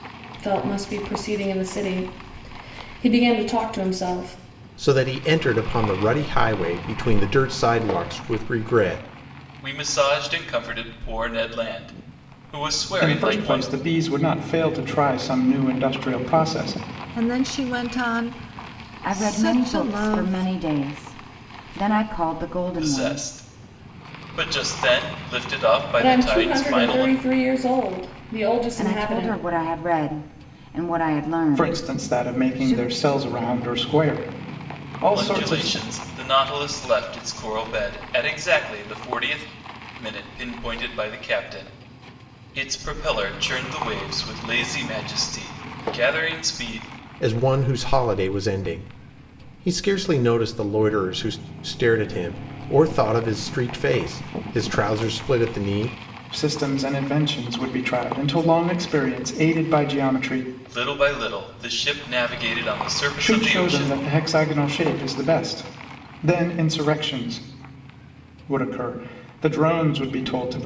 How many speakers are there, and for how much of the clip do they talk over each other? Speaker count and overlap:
six, about 10%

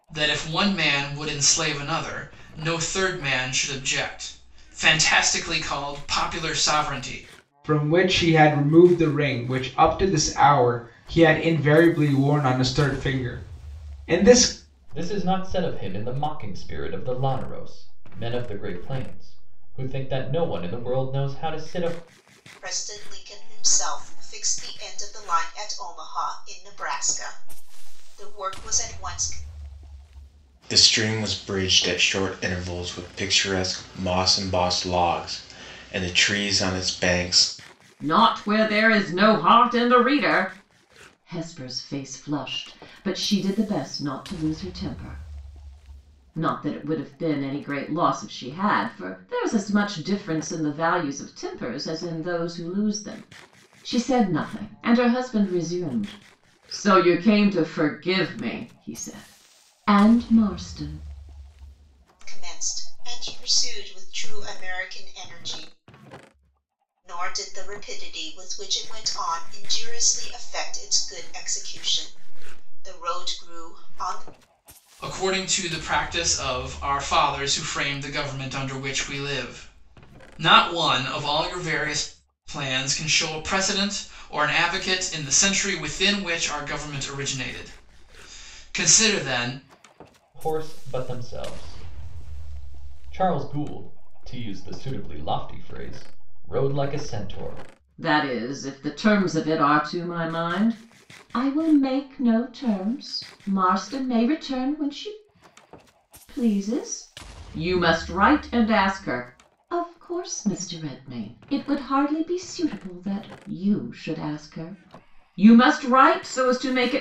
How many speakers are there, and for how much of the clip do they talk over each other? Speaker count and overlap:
six, no overlap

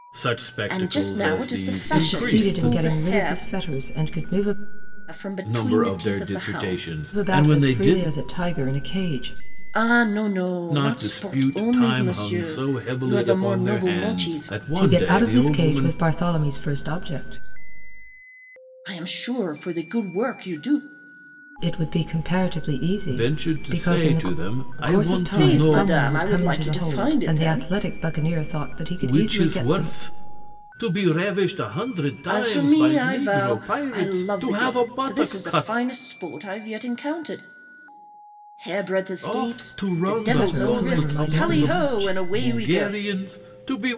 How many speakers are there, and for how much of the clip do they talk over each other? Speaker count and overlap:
three, about 51%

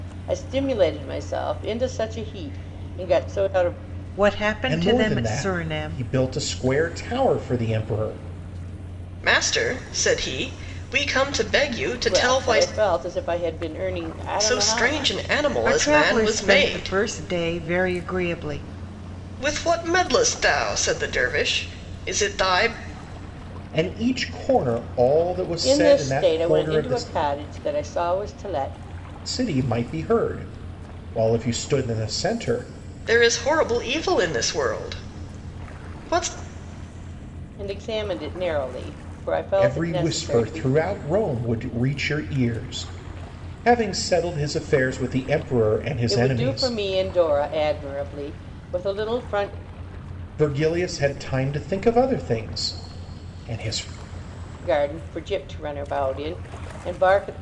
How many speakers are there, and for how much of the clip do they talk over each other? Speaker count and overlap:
four, about 13%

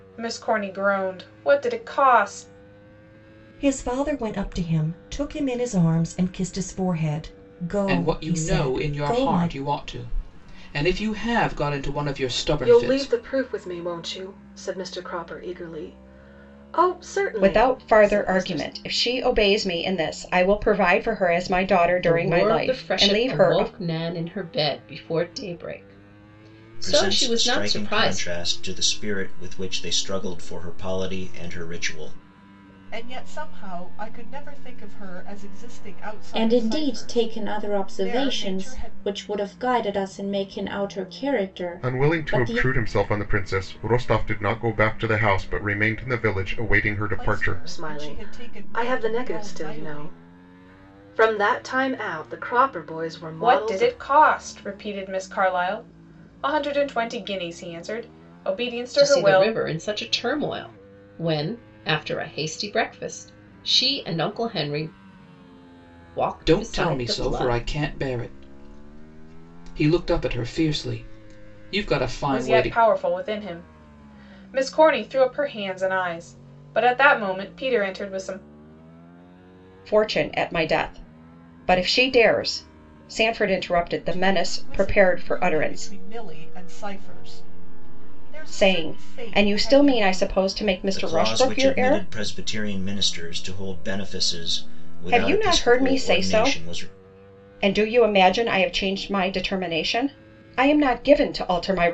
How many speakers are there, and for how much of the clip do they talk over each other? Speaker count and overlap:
ten, about 23%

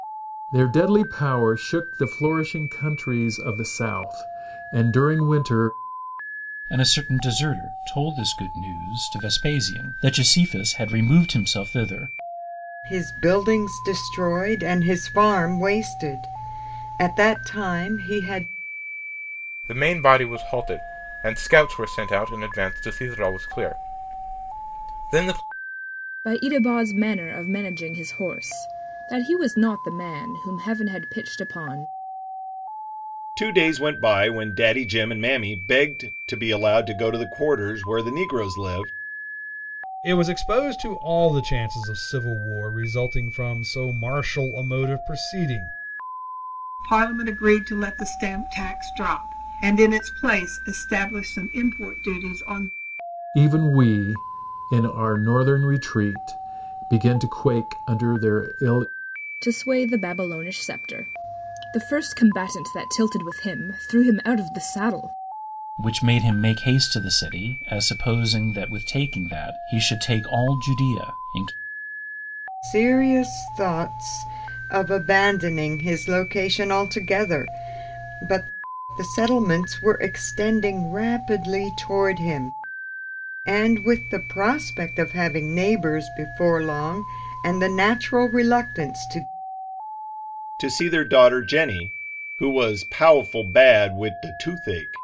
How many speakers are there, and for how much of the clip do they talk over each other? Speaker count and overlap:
eight, no overlap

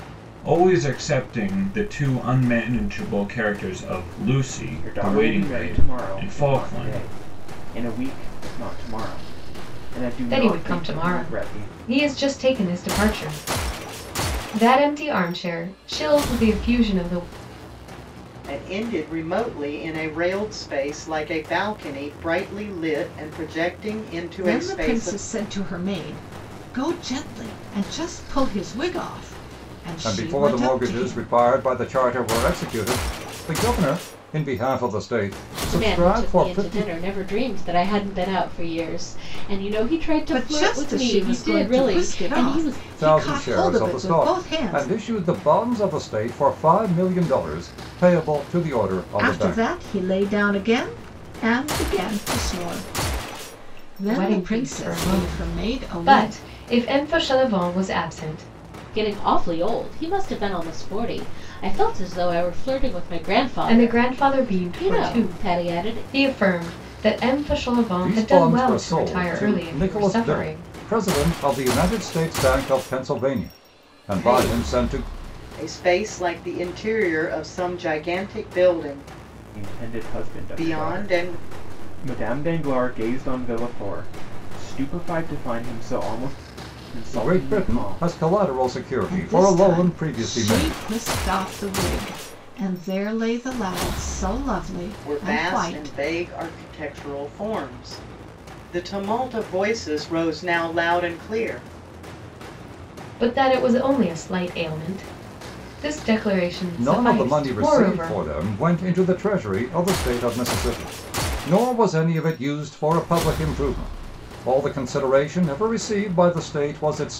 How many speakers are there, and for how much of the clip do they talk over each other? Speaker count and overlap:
seven, about 24%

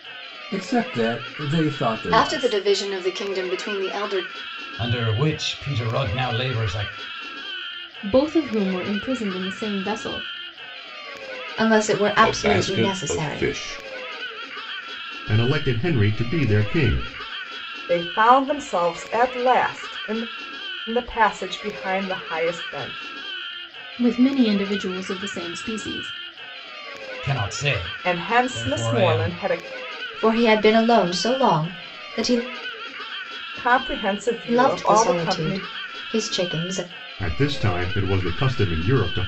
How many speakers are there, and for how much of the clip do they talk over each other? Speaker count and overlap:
eight, about 11%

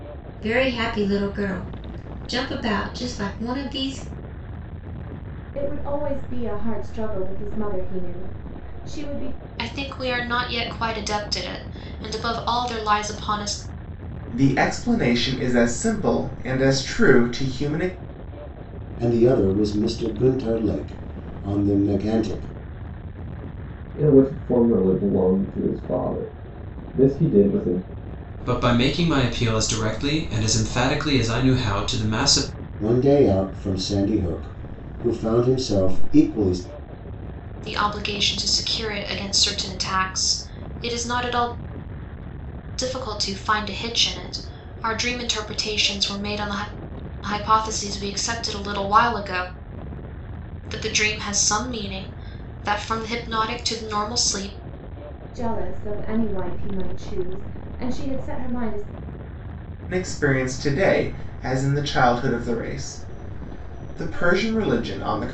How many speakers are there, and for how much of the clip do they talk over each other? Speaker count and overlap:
seven, no overlap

